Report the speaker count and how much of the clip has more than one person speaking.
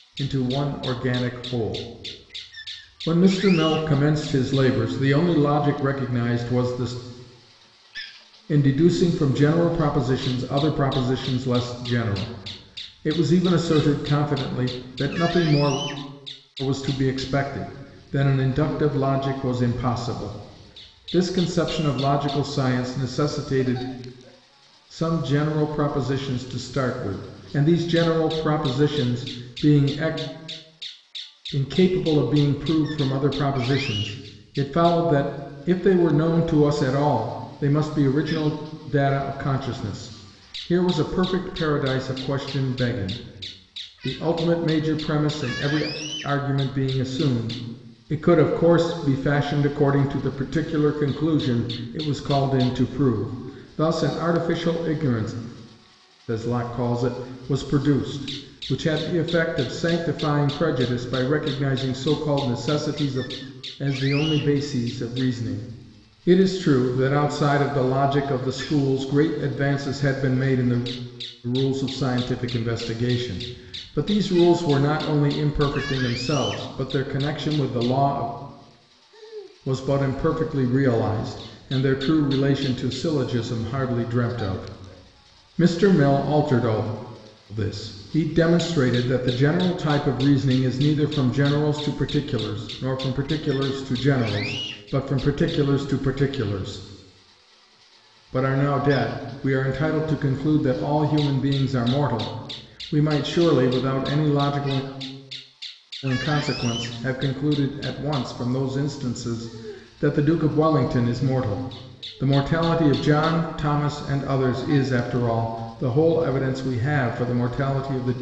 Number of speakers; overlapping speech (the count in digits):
1, no overlap